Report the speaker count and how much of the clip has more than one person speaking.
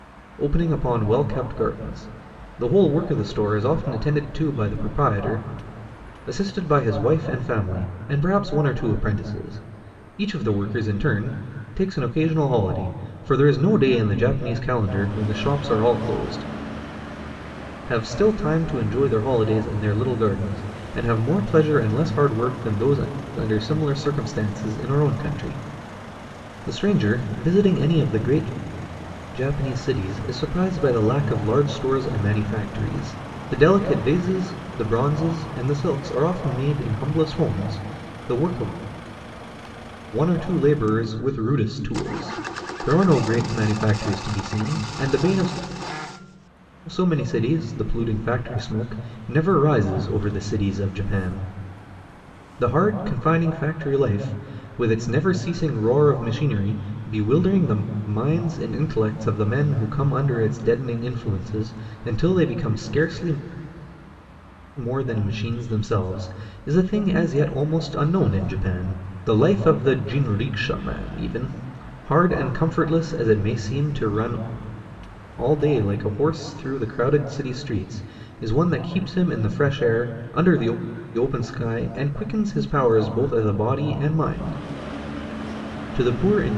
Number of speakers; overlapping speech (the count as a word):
one, no overlap